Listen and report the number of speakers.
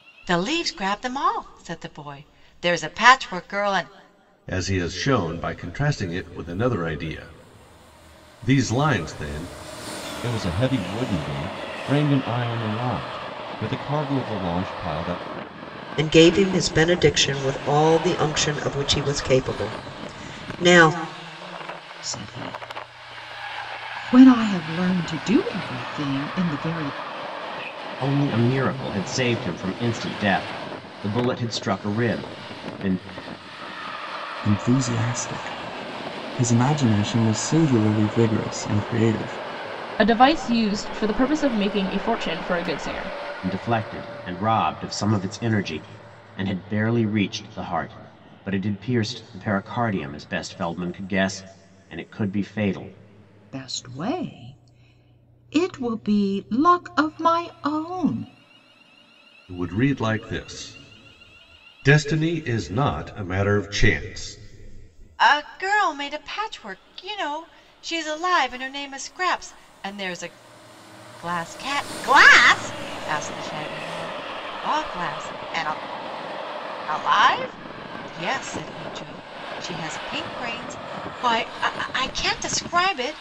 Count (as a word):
eight